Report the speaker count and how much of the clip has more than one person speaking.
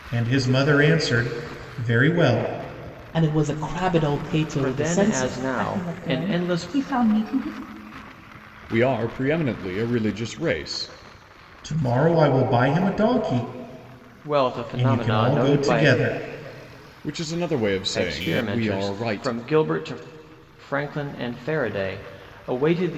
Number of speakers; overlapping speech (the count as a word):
five, about 20%